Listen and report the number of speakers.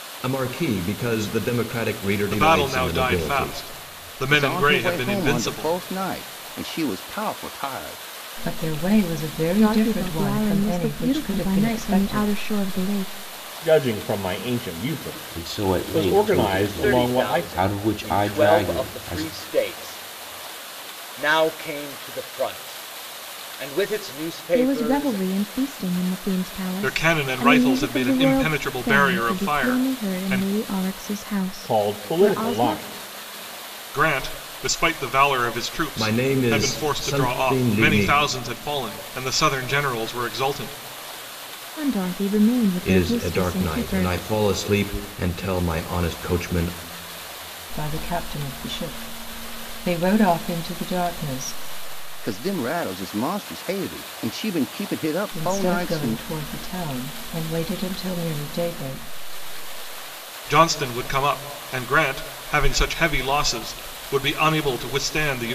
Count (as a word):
eight